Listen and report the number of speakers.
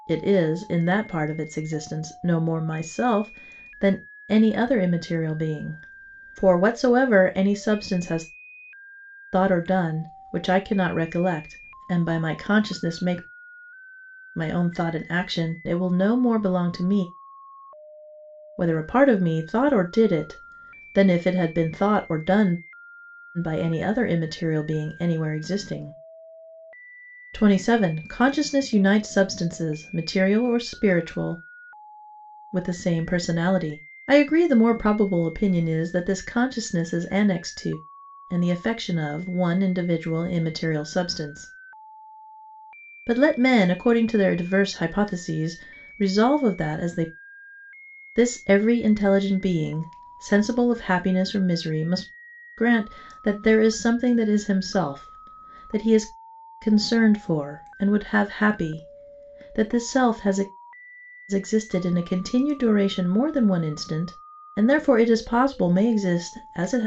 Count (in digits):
1